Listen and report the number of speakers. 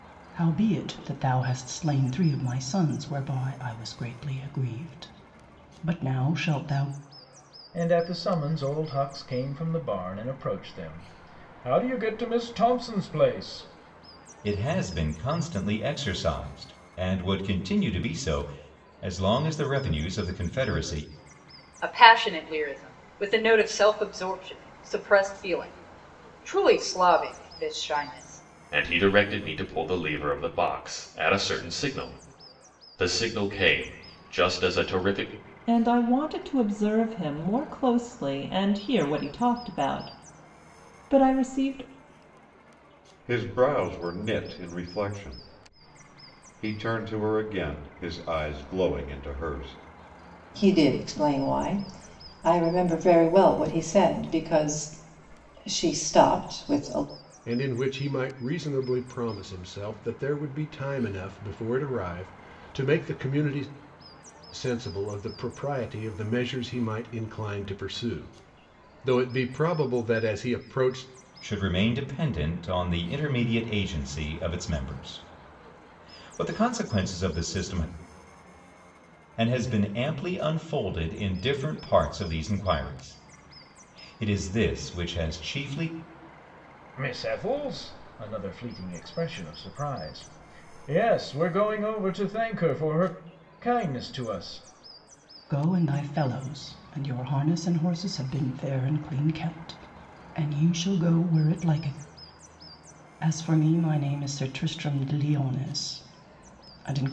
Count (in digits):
9